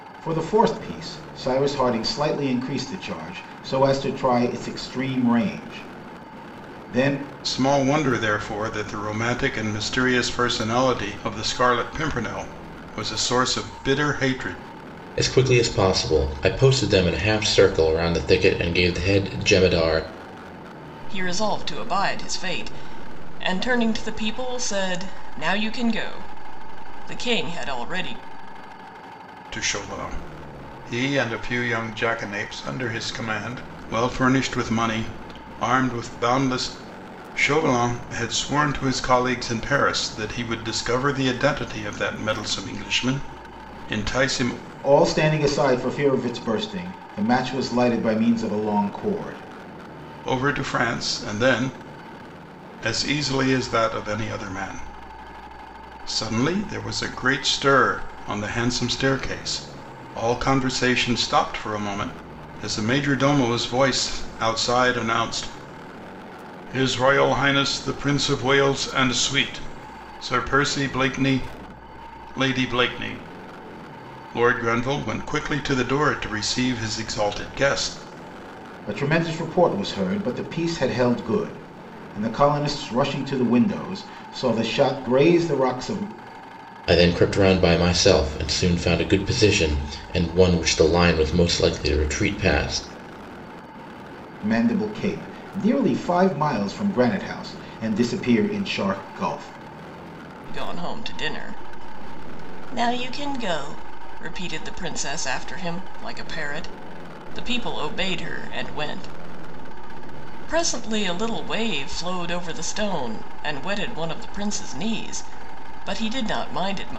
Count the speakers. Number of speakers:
four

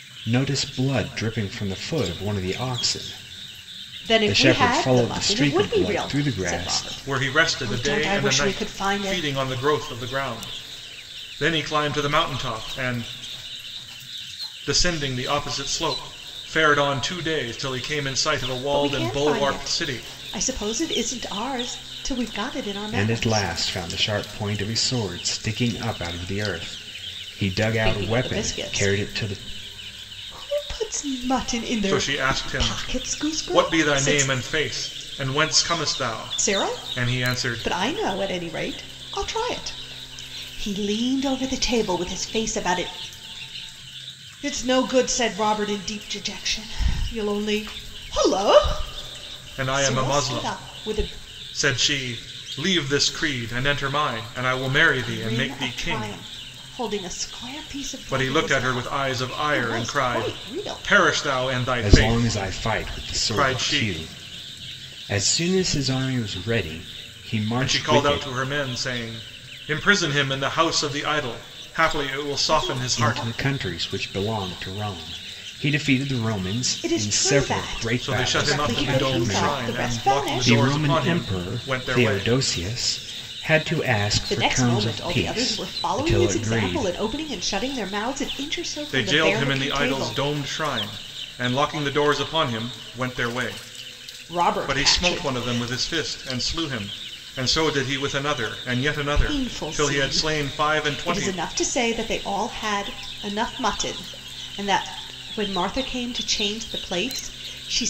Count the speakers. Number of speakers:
three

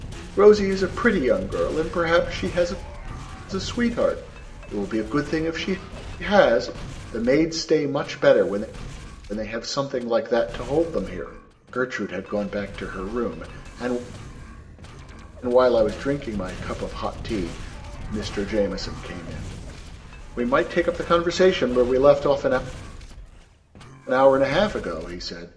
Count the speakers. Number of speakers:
one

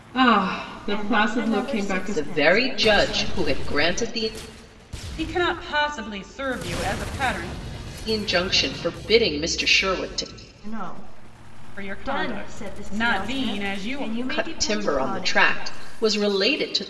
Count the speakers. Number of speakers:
four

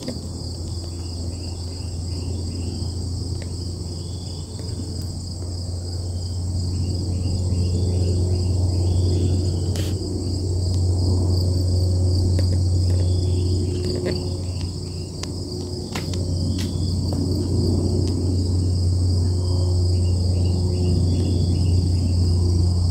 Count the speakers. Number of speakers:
zero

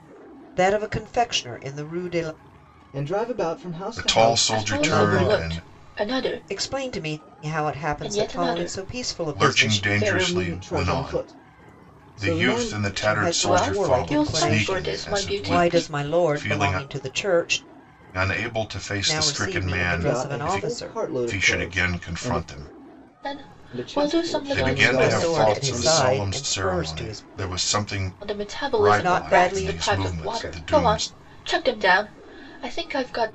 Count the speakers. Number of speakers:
four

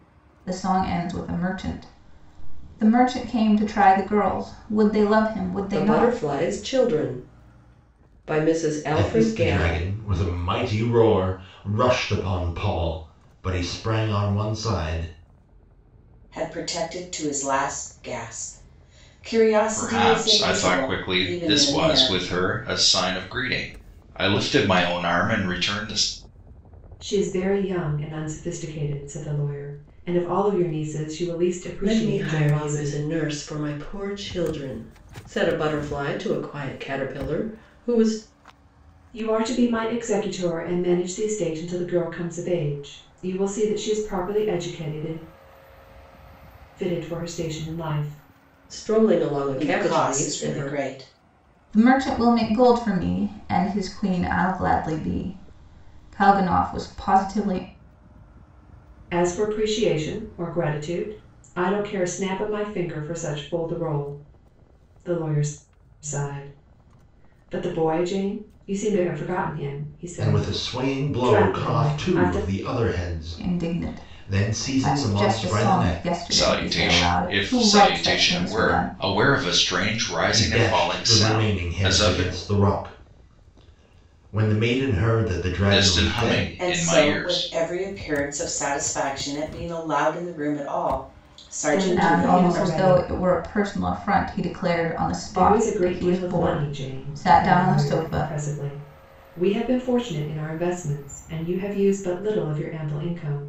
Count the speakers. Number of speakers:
six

